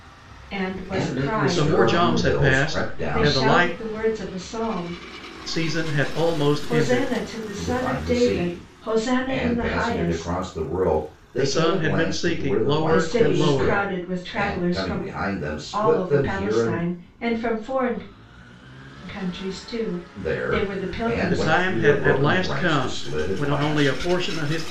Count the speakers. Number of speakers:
3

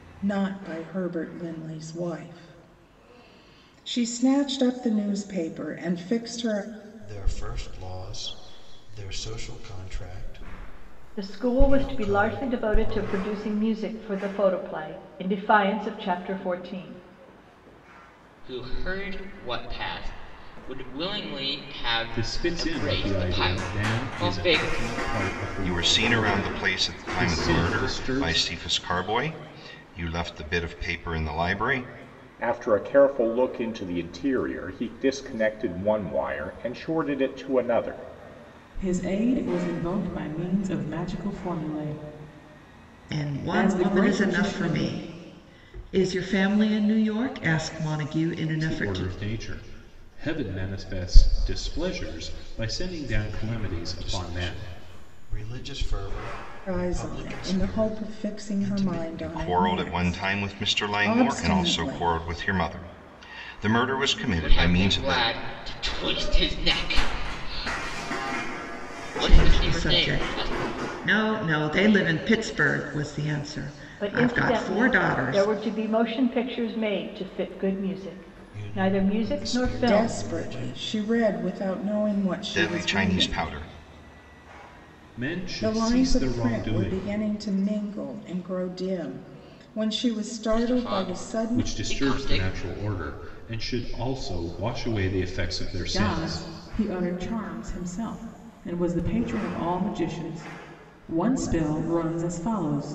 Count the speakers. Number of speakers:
9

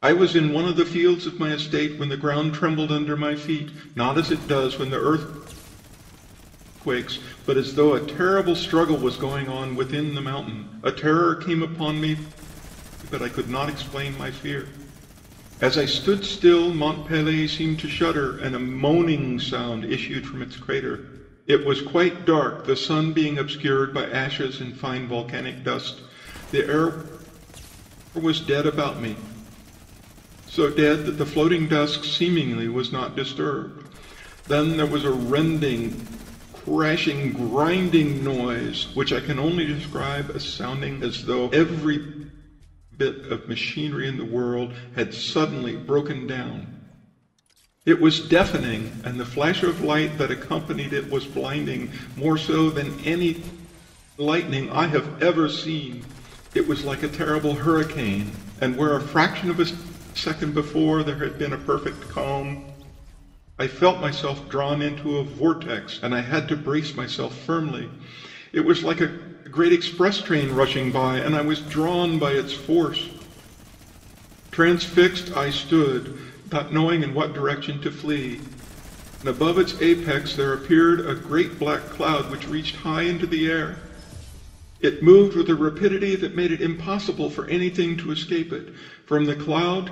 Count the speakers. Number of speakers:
1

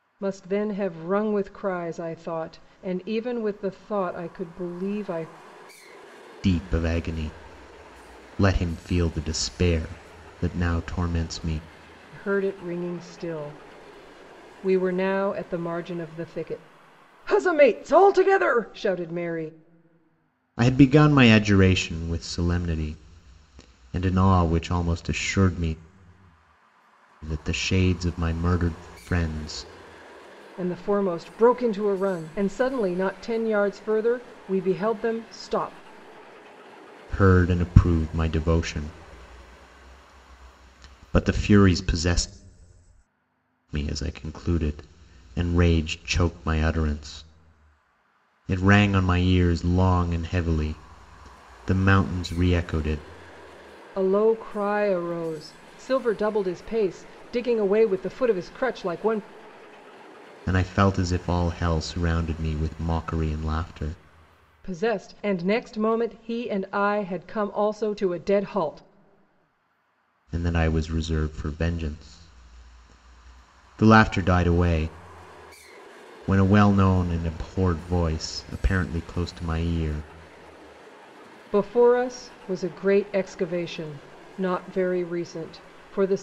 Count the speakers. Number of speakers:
2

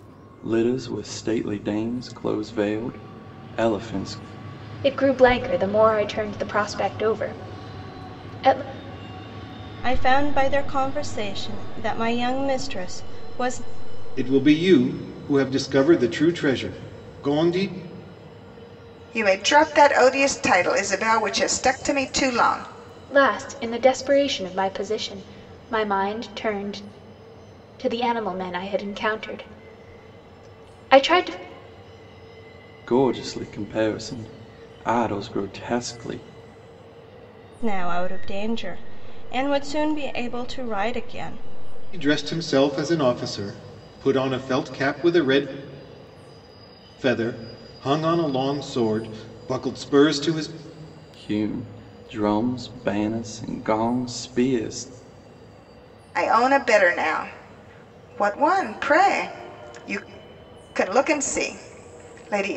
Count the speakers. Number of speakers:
5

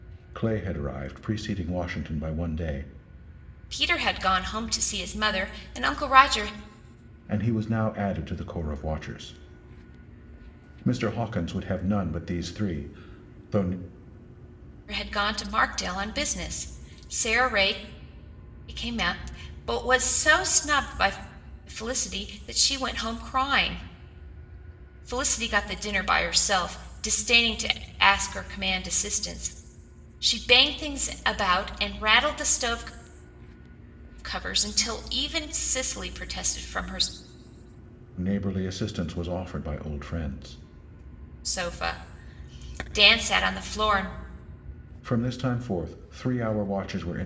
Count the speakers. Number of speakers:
2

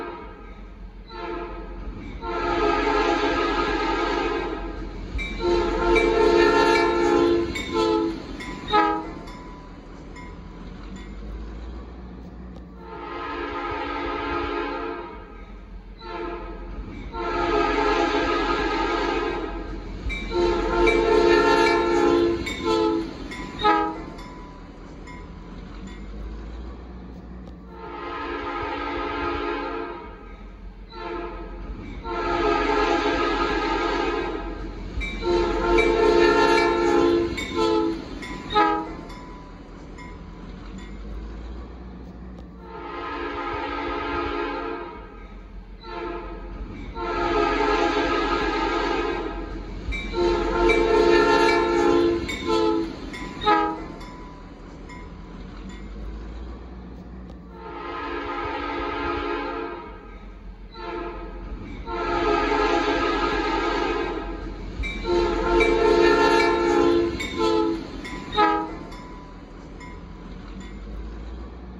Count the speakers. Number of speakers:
0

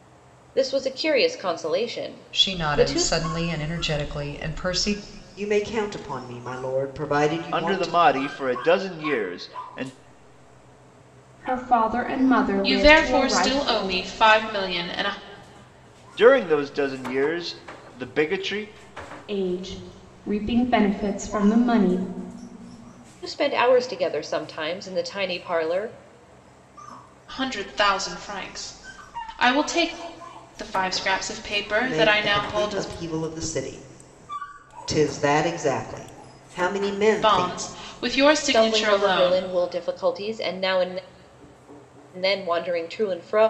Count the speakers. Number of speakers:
6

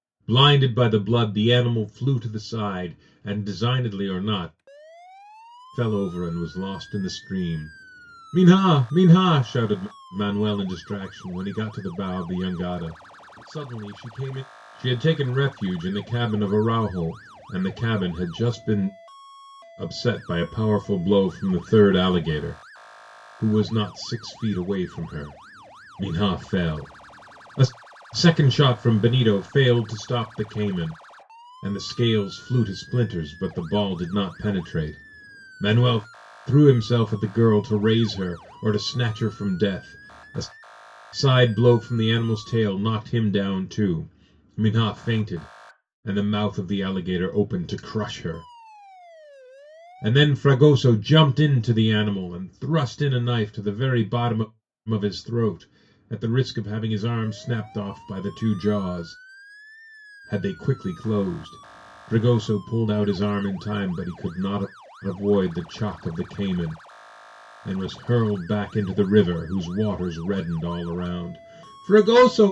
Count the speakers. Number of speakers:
1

